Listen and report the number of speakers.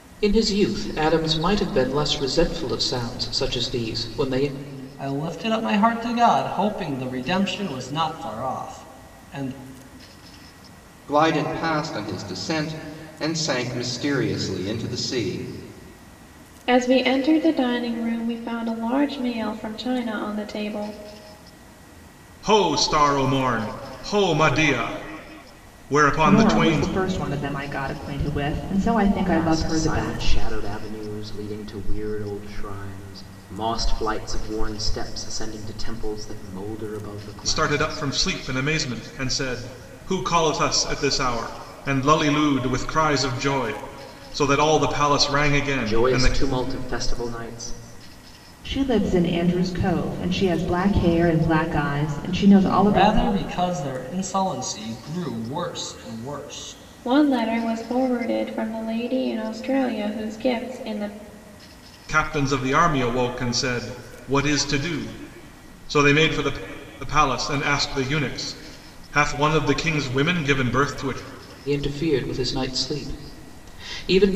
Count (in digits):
7